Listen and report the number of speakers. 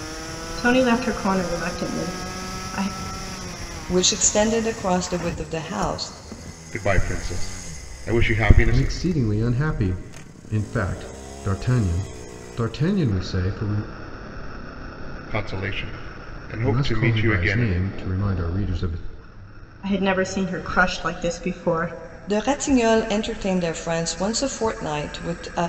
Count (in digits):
4